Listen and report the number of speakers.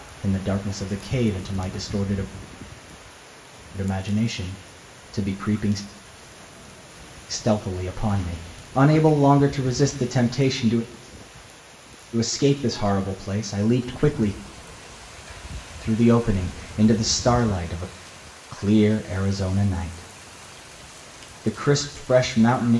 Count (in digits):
1